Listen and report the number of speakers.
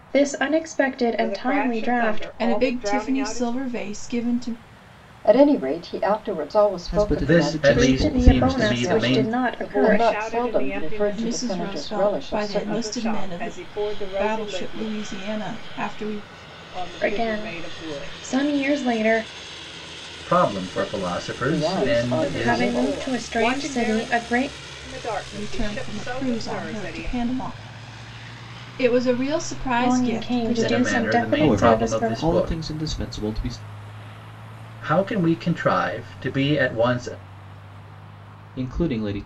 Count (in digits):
6